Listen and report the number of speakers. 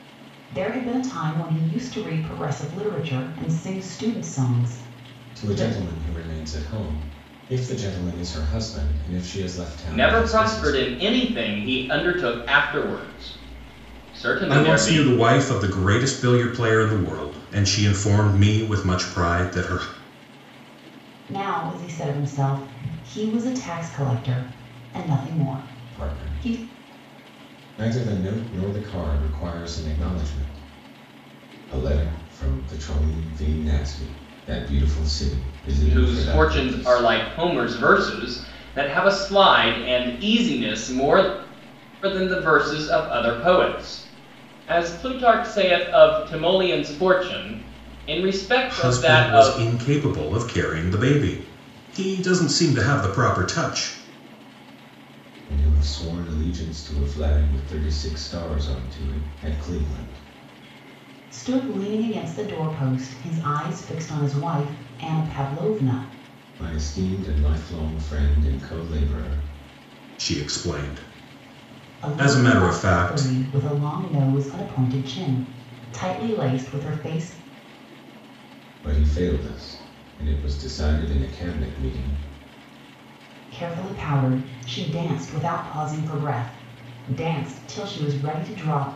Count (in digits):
4